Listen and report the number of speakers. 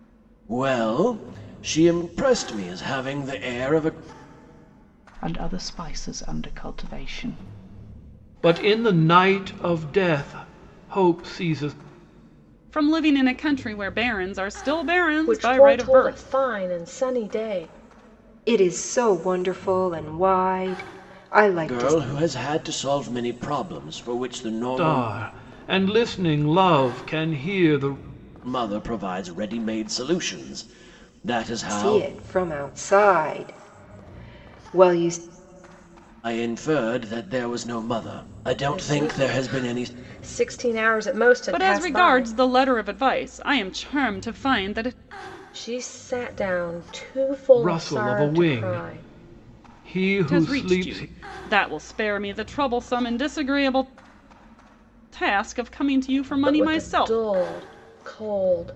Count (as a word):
six